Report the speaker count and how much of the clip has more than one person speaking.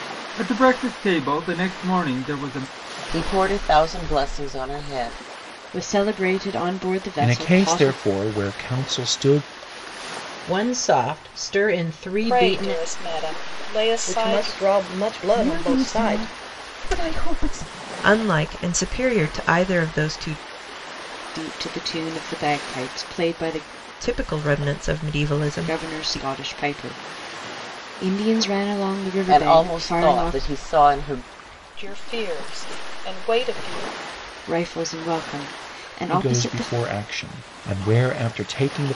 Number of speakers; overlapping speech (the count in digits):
9, about 15%